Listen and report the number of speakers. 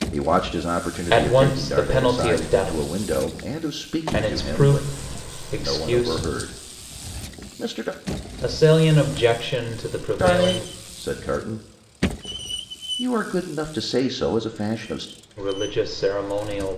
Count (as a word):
two